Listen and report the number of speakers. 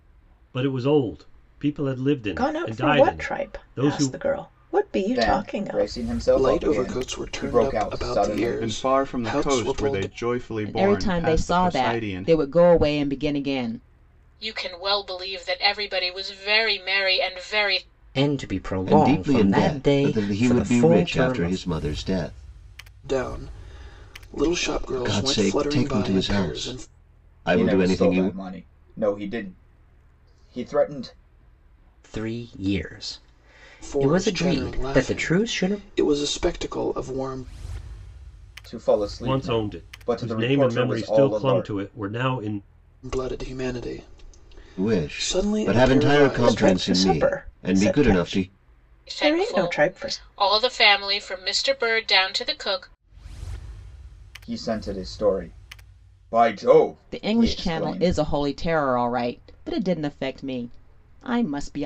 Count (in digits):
9